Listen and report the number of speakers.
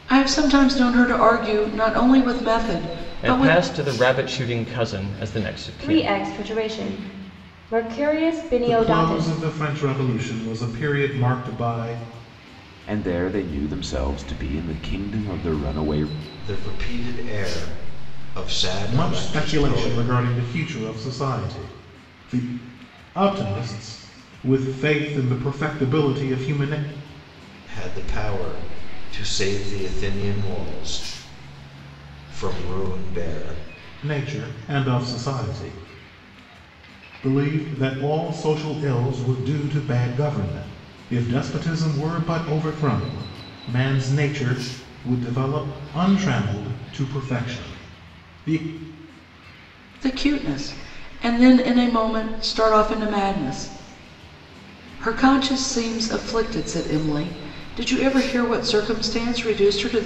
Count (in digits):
6